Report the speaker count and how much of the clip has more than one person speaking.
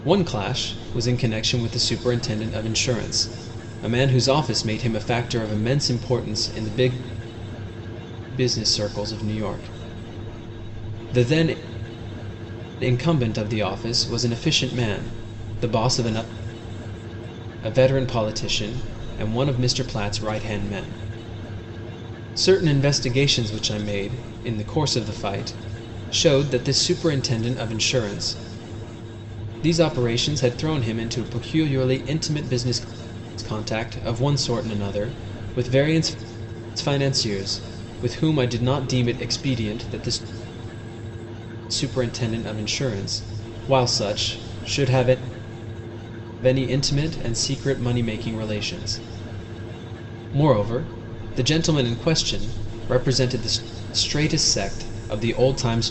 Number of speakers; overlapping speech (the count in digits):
1, no overlap